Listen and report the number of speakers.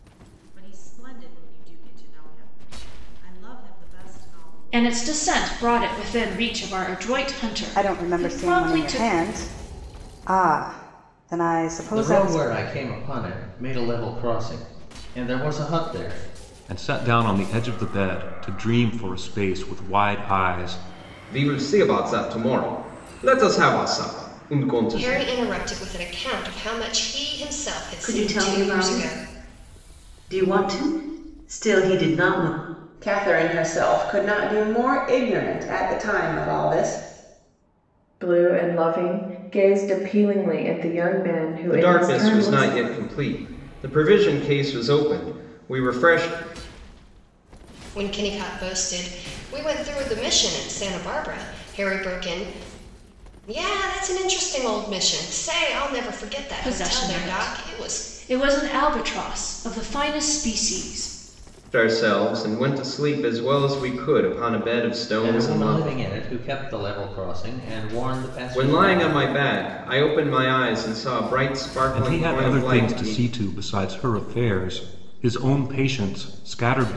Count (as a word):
ten